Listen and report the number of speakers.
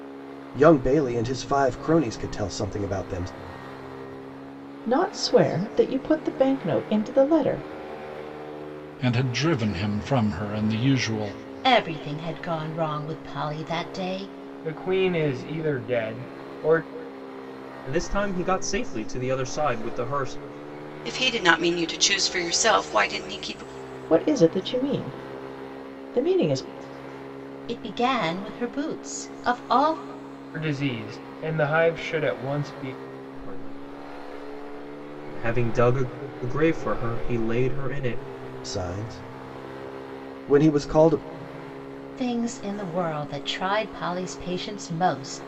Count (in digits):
7